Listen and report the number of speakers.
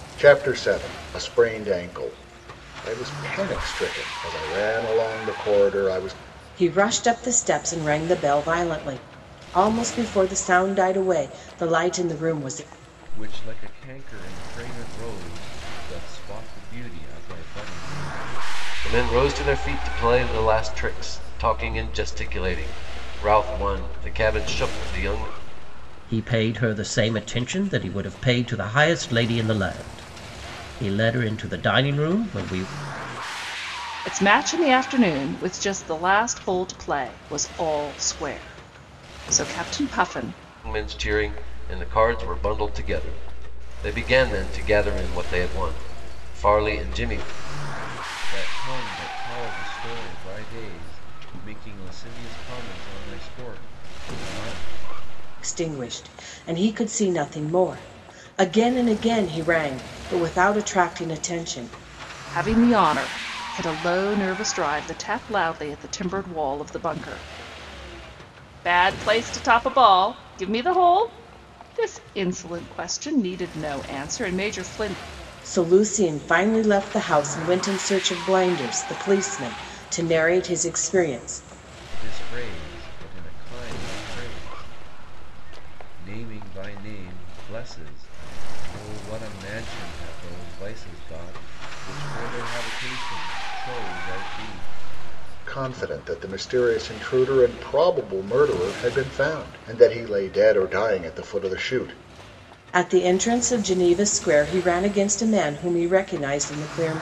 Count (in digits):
6